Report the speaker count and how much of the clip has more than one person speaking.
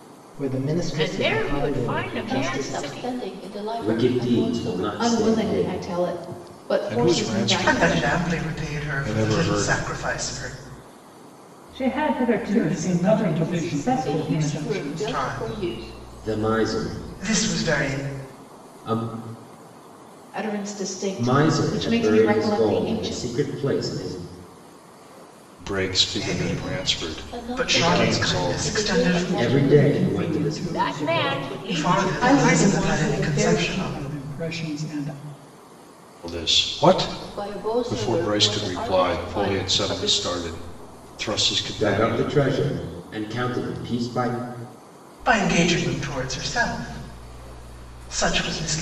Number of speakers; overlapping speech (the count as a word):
nine, about 53%